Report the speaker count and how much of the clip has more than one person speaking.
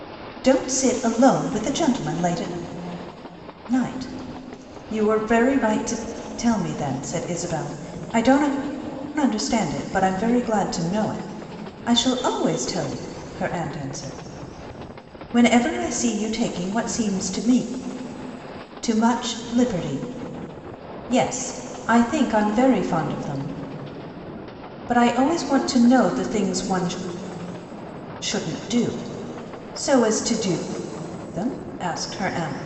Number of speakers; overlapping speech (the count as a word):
one, no overlap